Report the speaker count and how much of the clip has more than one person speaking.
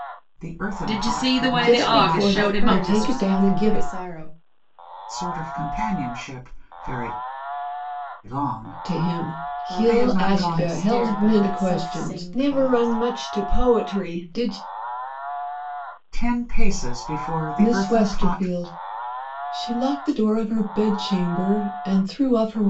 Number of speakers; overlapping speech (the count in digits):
4, about 37%